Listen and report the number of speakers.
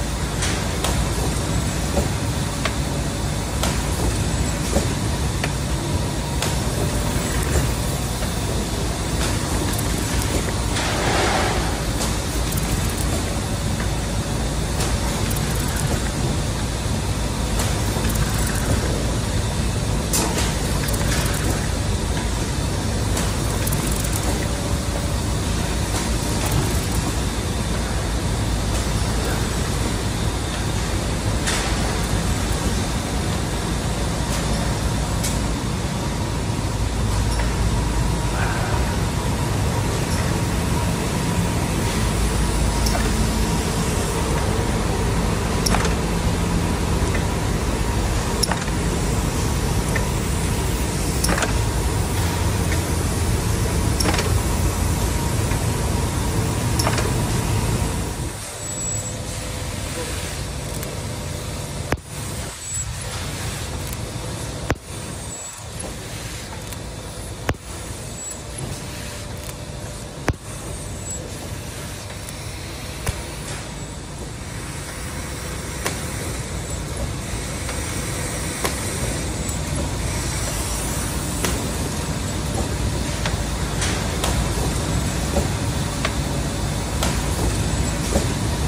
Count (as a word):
zero